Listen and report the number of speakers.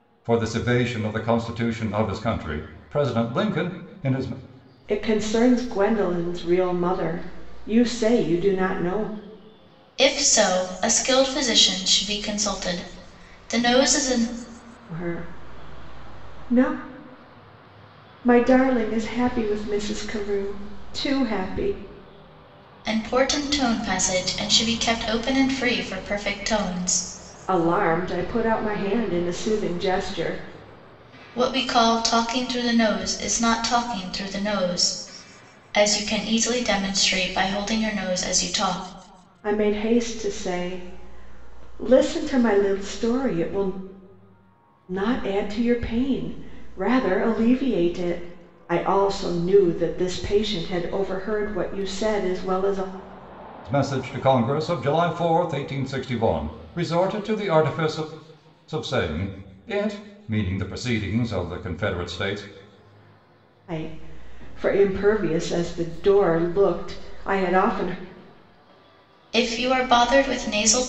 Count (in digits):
3